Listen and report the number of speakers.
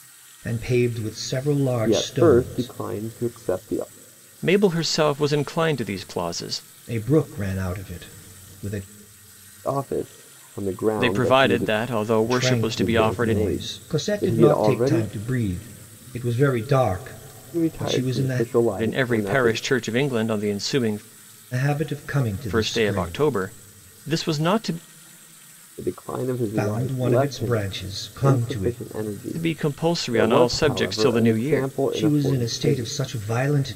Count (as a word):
three